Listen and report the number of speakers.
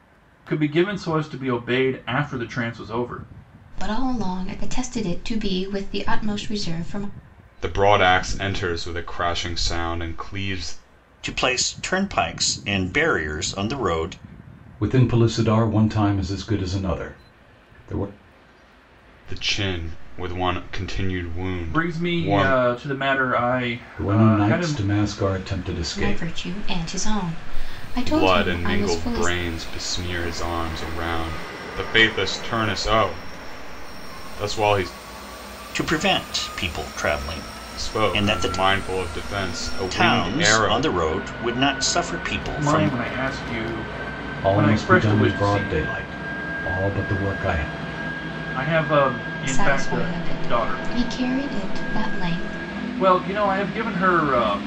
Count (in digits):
5